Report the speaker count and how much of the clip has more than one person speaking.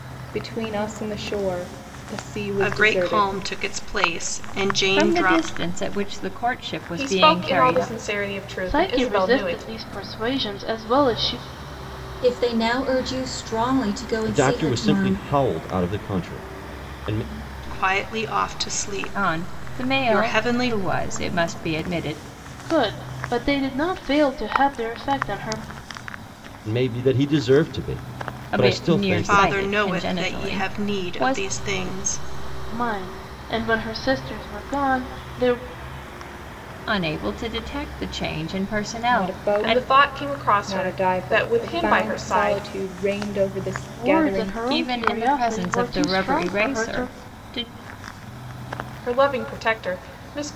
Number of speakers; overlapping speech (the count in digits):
7, about 31%